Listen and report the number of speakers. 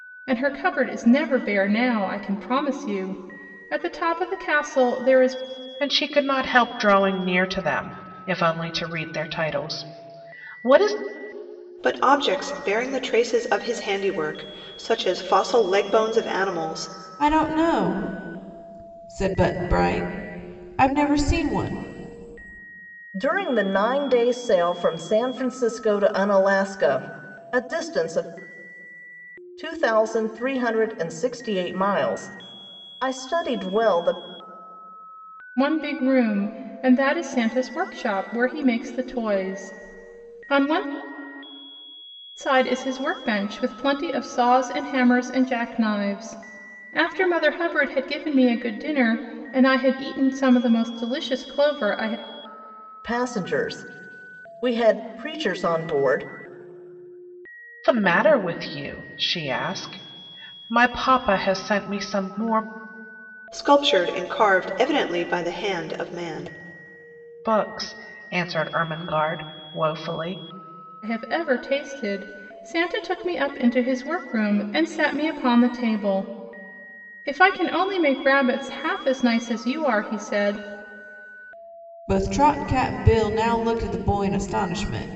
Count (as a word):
five